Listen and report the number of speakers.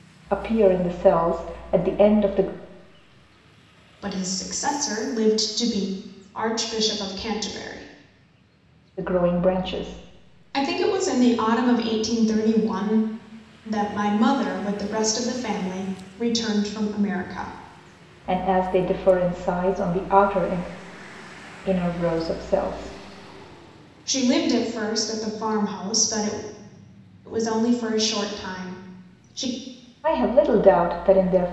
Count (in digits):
2